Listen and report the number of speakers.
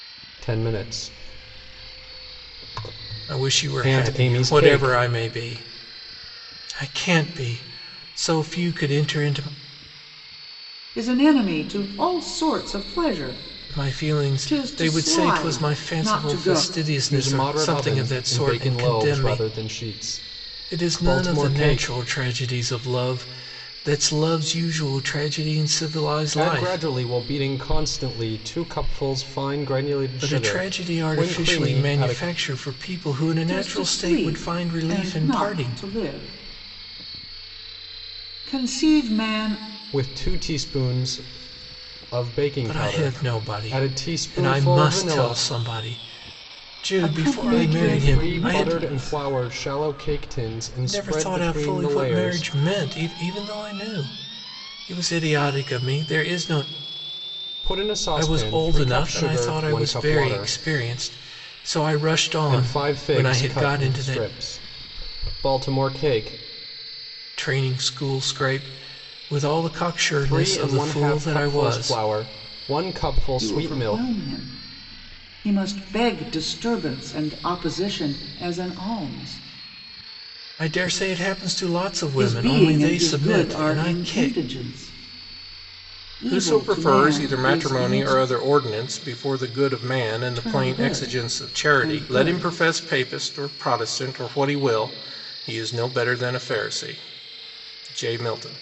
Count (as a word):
three